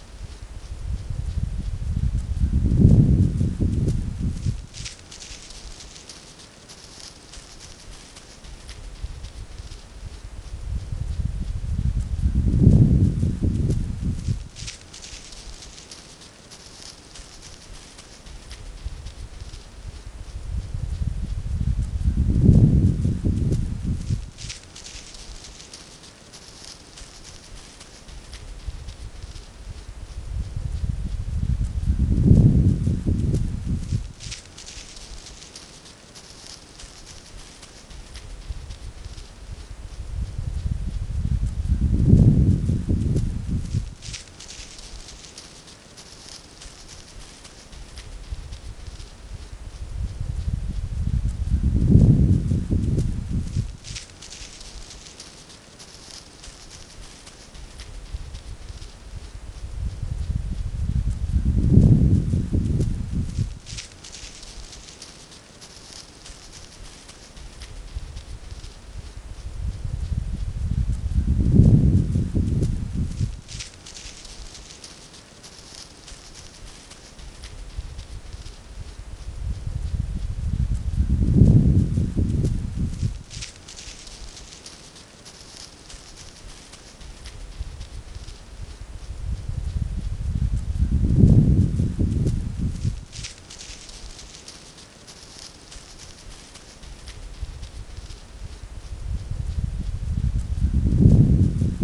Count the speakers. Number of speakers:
0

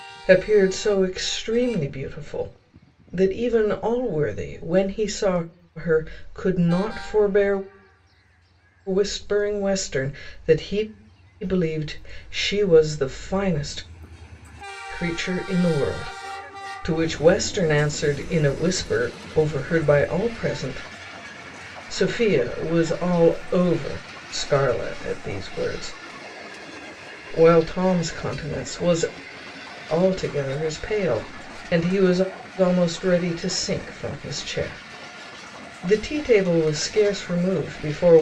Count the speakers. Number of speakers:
1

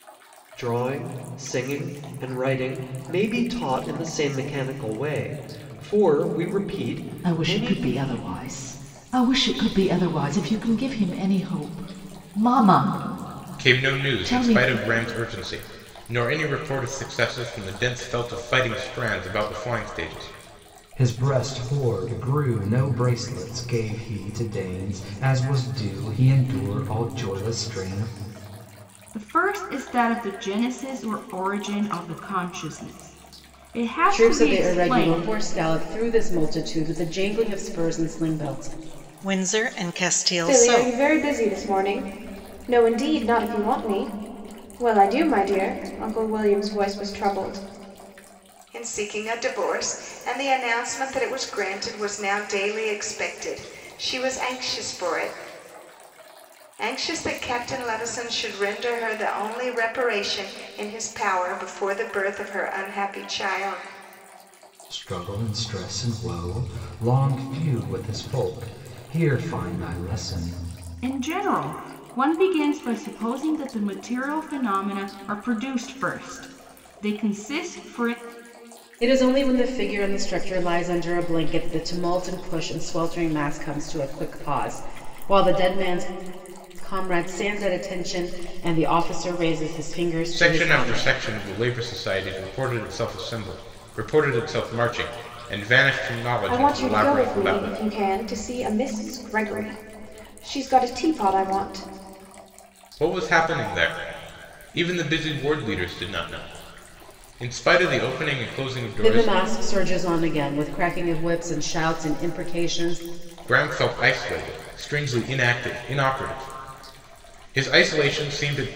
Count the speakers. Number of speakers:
9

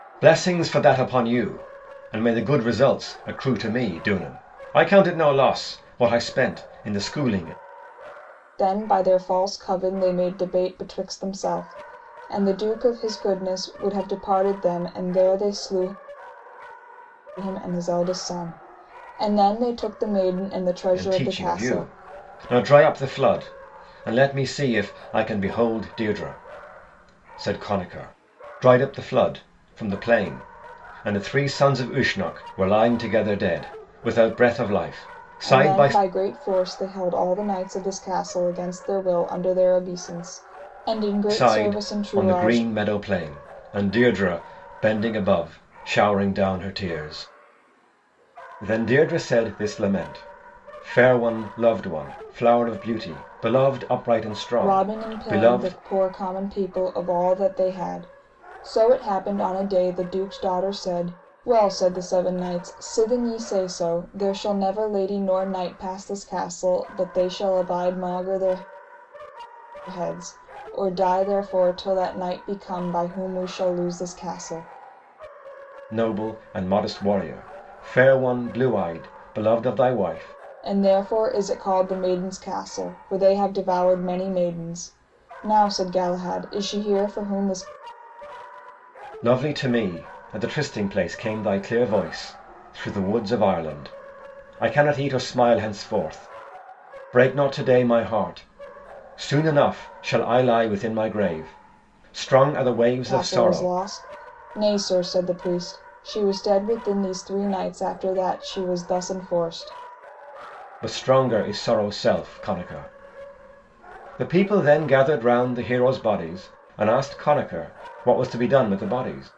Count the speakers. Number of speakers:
2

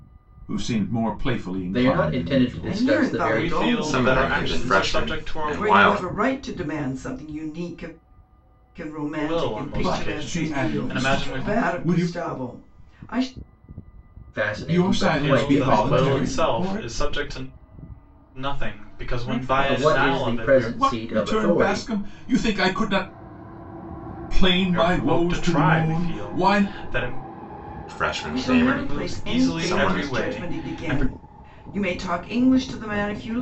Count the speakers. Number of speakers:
5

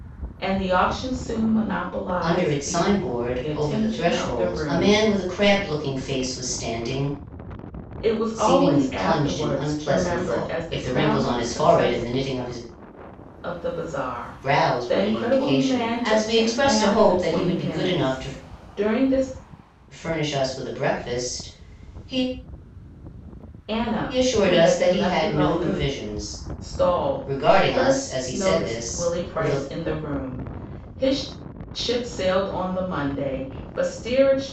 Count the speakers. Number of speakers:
2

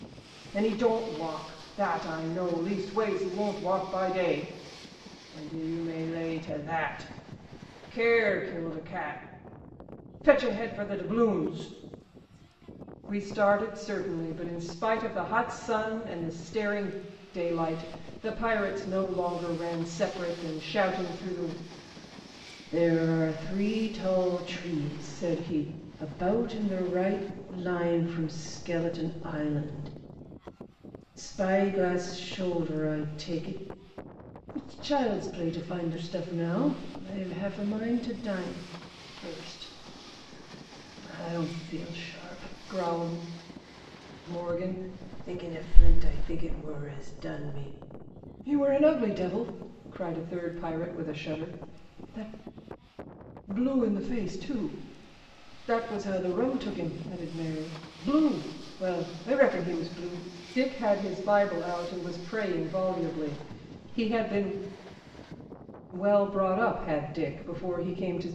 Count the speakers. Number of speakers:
1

